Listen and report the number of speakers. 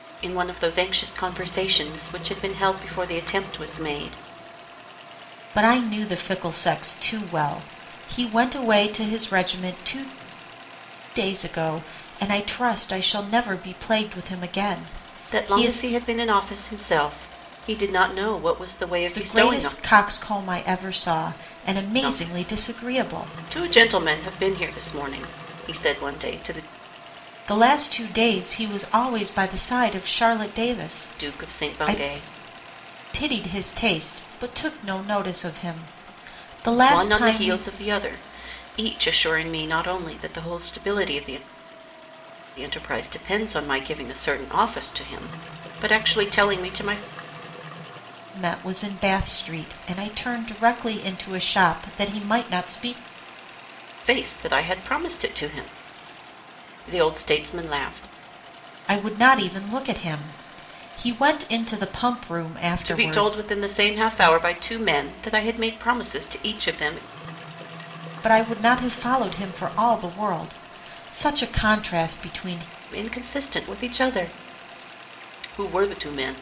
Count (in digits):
2